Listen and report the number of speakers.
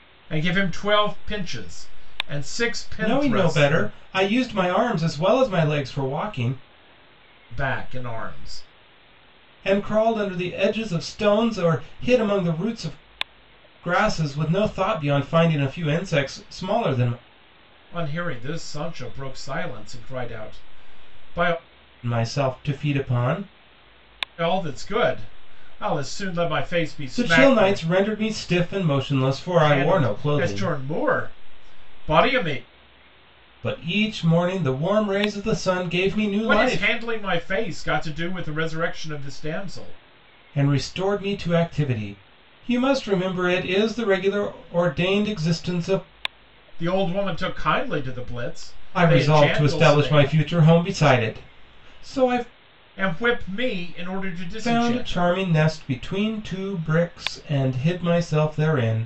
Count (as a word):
two